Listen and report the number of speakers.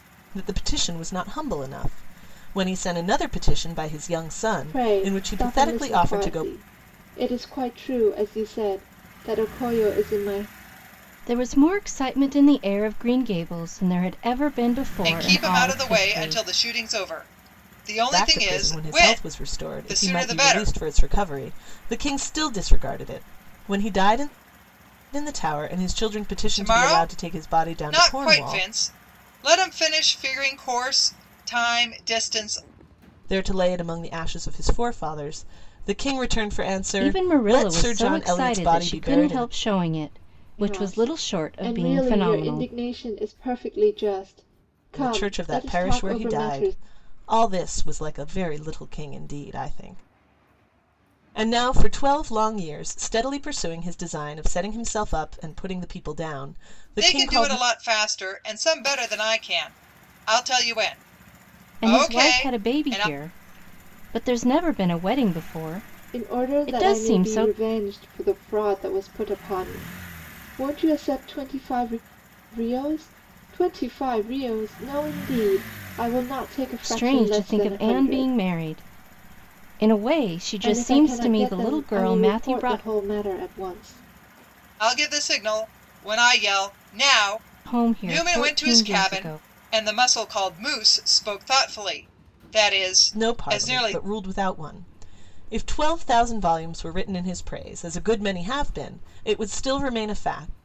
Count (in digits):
4